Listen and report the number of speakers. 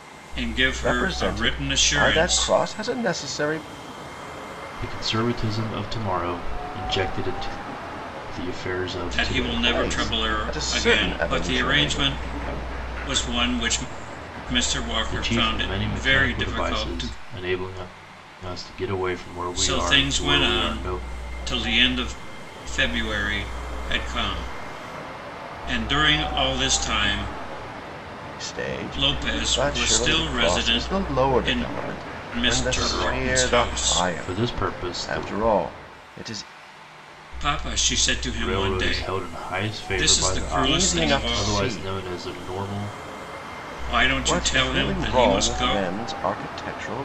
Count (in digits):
3